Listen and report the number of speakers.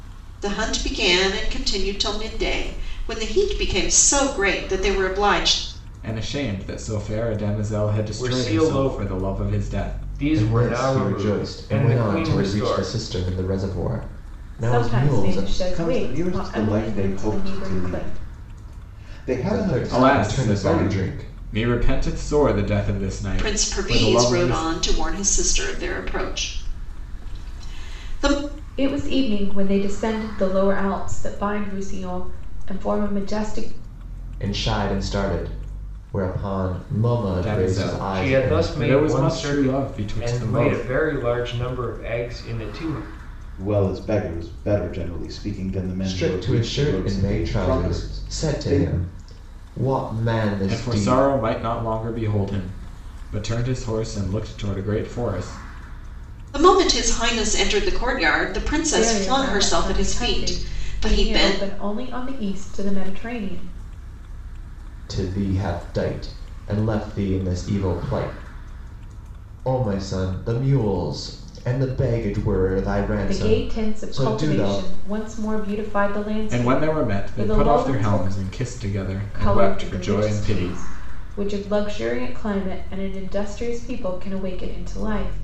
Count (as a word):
six